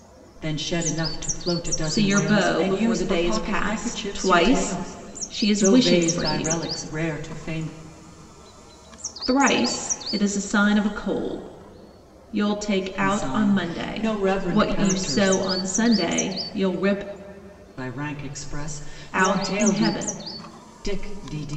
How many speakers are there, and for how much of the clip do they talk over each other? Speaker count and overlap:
two, about 35%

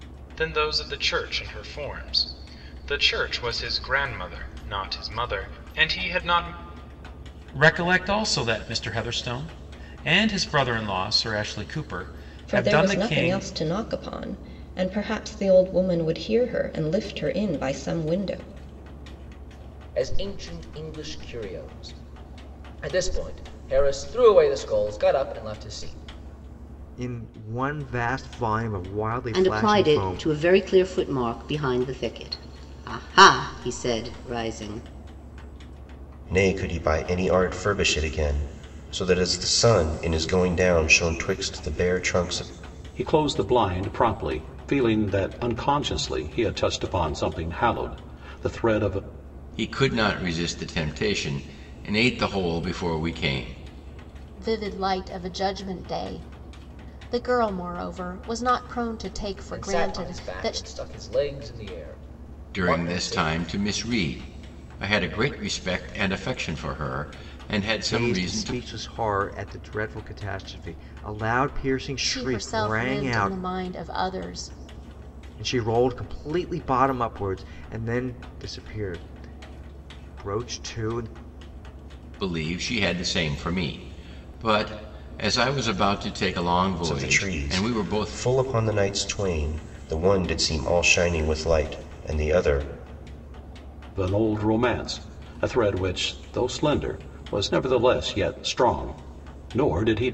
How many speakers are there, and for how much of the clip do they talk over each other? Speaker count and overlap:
ten, about 8%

